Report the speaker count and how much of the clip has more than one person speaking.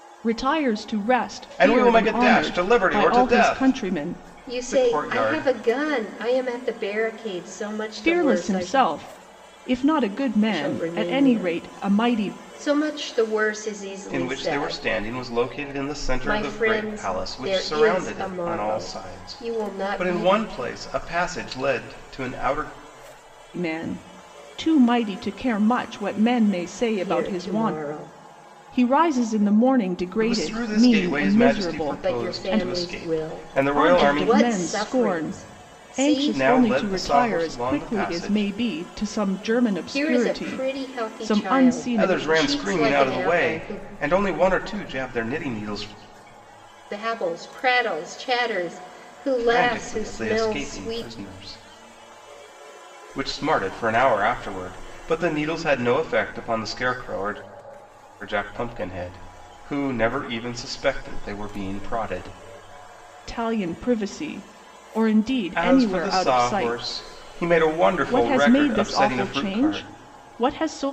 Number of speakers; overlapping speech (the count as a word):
three, about 42%